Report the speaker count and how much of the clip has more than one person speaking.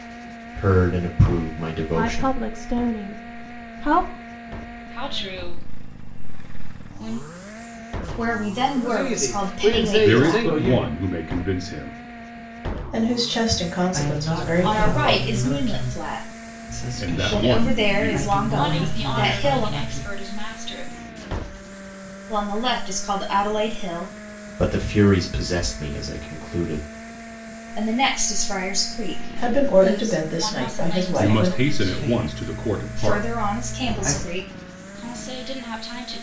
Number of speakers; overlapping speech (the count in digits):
8, about 36%